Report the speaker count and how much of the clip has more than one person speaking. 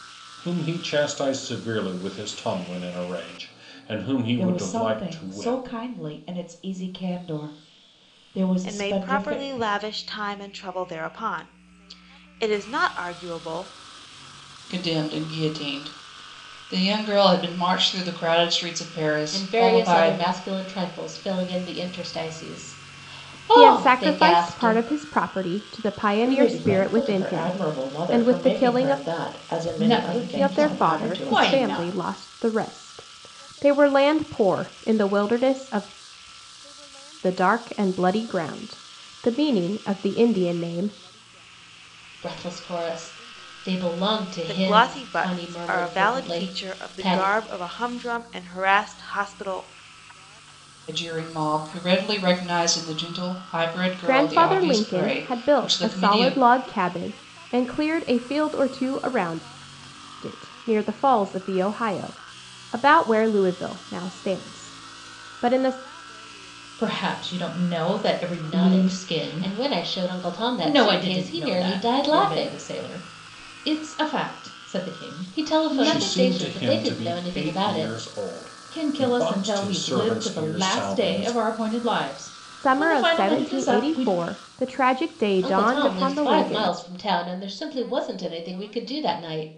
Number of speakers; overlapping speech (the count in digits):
8, about 30%